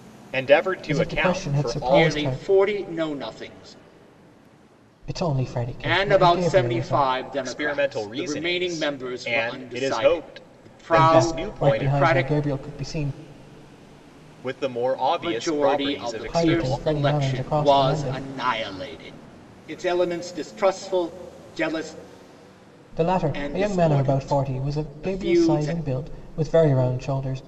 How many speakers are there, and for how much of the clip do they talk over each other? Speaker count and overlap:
3, about 48%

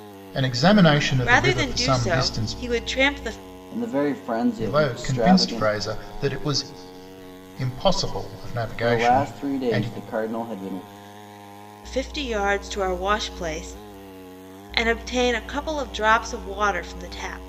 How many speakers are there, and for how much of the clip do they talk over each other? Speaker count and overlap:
3, about 23%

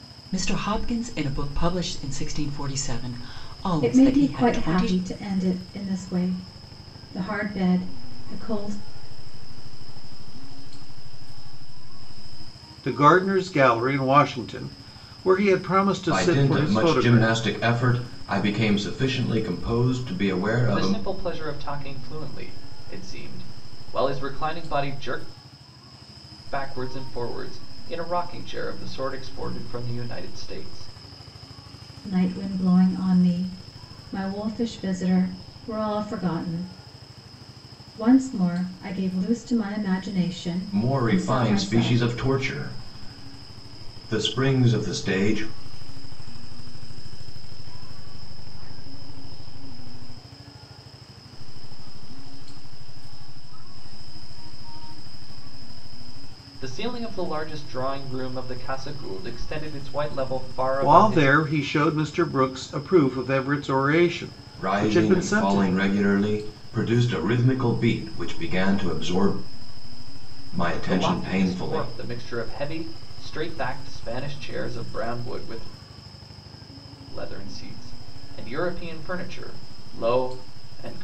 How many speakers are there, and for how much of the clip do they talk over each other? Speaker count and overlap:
6, about 12%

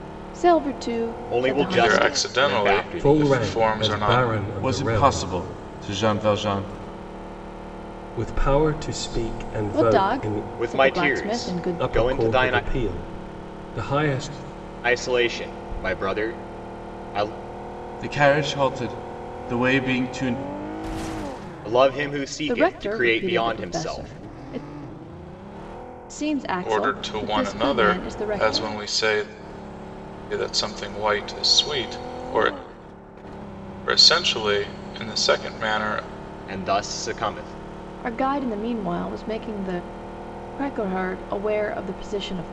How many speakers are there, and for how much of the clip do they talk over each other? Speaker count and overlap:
5, about 25%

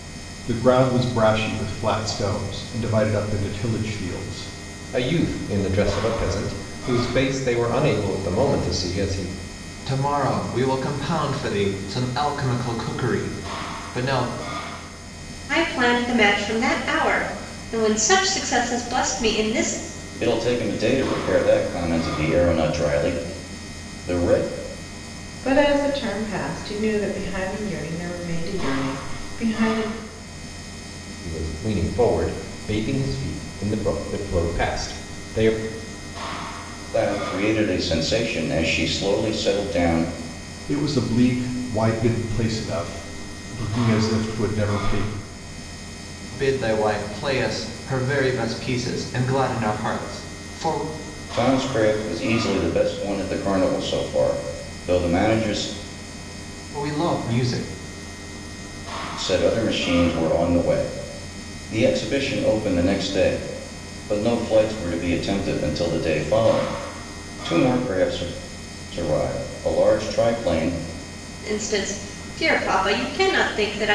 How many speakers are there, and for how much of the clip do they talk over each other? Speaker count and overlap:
6, no overlap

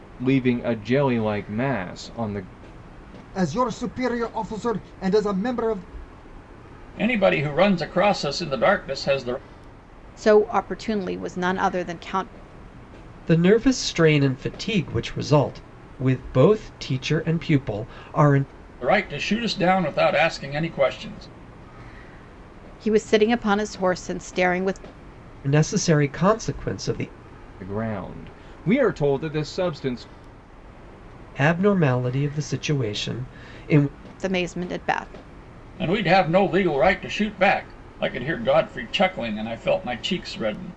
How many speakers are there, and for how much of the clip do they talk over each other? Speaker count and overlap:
5, no overlap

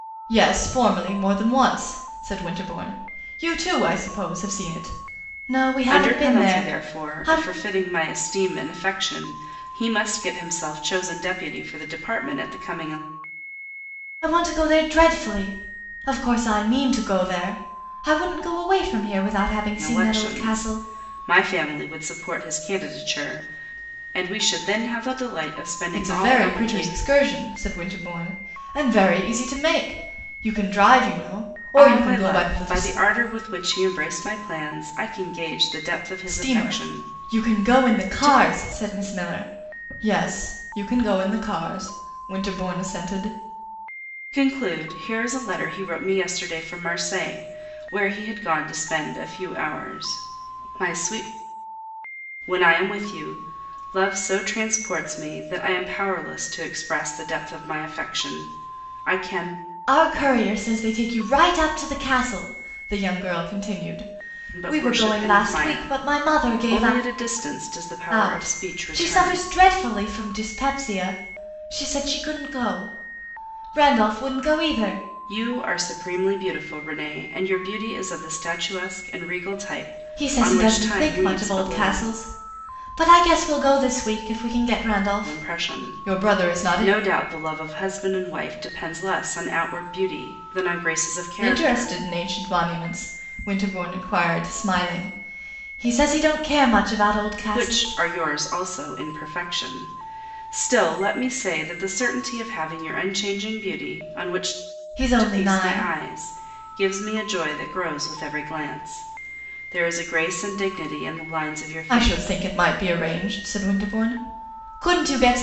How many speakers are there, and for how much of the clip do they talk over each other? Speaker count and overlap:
2, about 14%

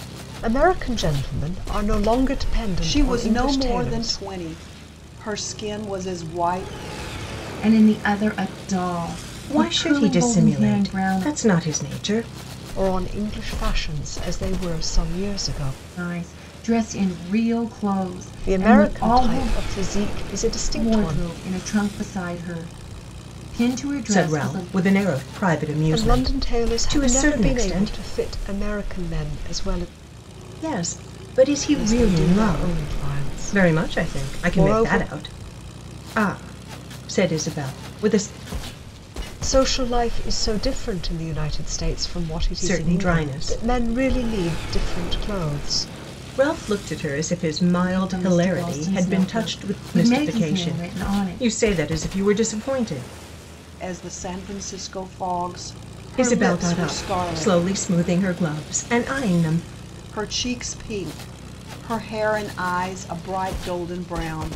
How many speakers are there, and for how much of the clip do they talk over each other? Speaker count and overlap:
4, about 27%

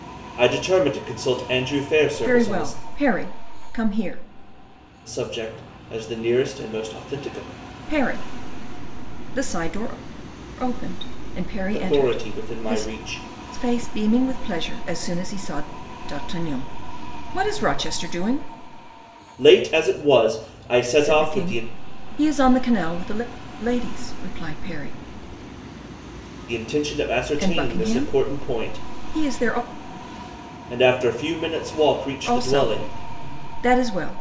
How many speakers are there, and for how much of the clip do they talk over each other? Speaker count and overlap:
2, about 14%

